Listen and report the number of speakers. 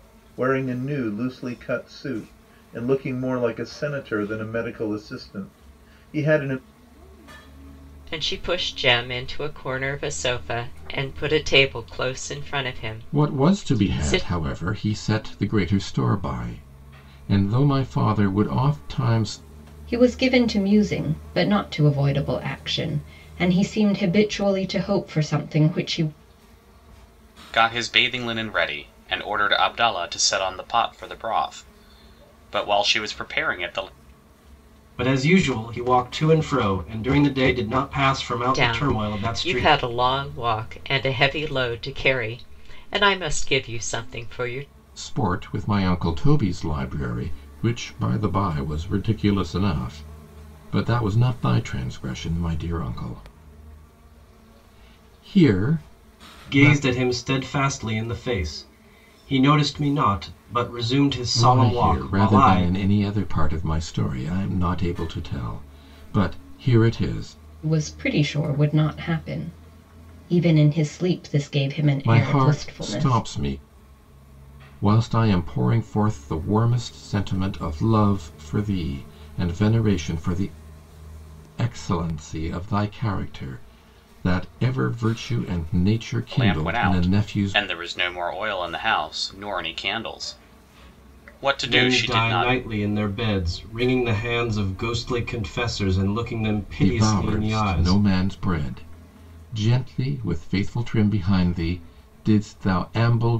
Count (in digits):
6